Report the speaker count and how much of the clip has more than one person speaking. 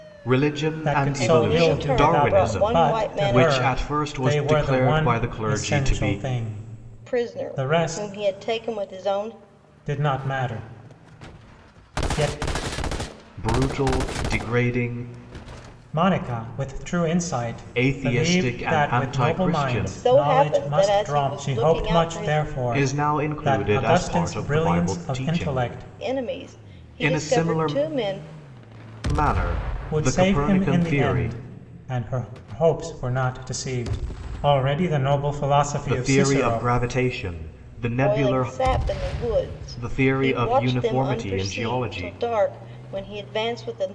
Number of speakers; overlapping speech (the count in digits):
3, about 48%